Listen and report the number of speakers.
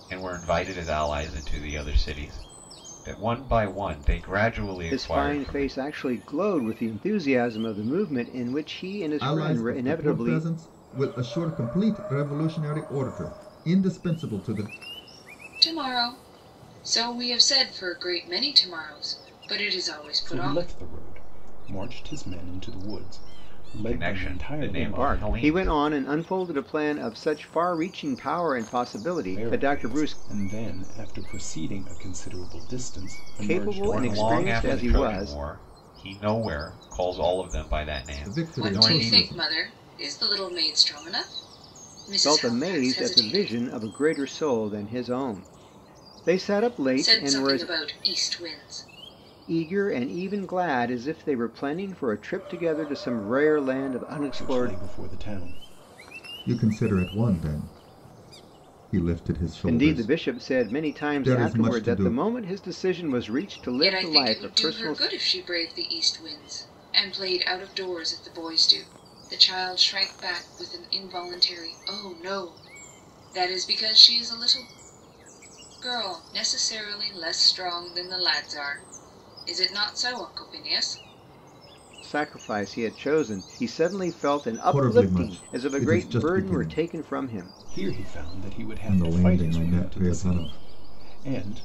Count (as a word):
five